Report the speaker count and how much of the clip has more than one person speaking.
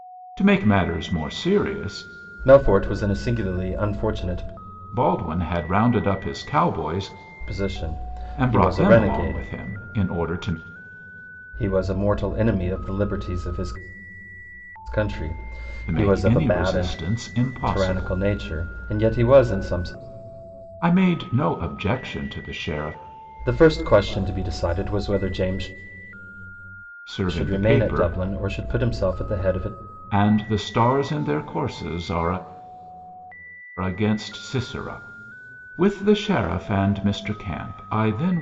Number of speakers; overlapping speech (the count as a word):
two, about 10%